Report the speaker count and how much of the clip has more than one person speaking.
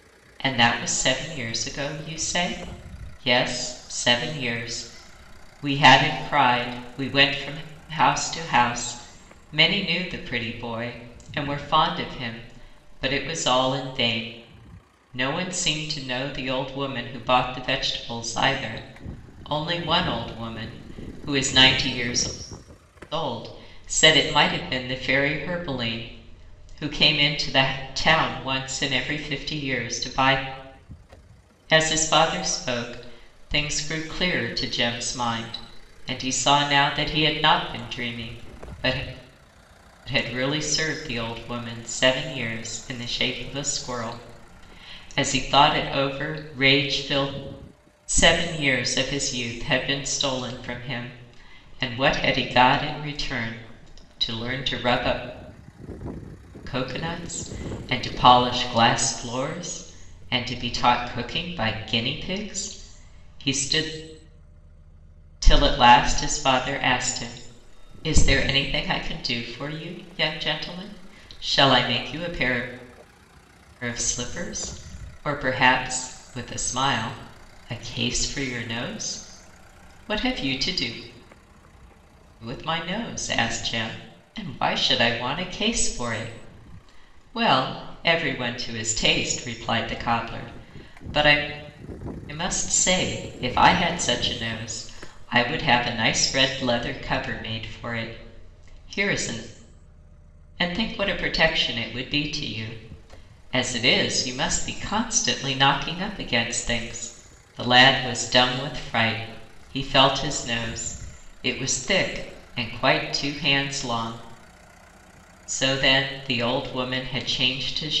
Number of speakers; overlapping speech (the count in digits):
1, no overlap